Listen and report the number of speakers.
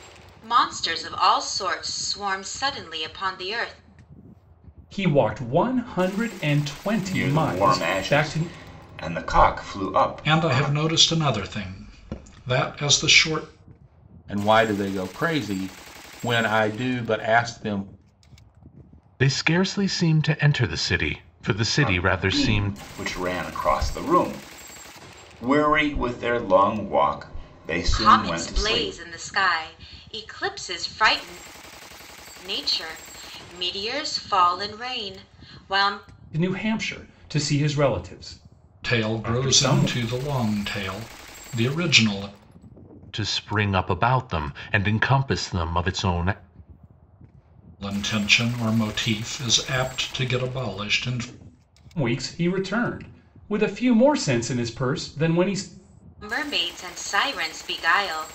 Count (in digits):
6